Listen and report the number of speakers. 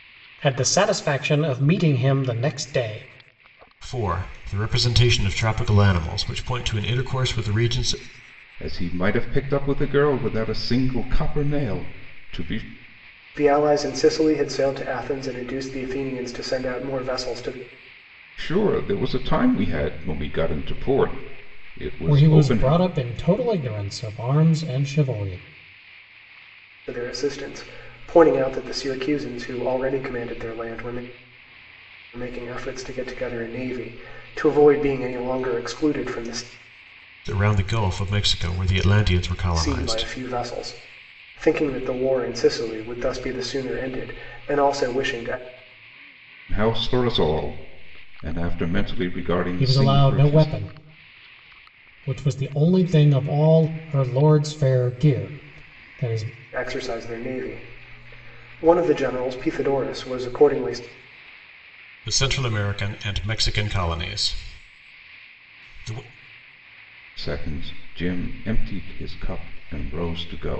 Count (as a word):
four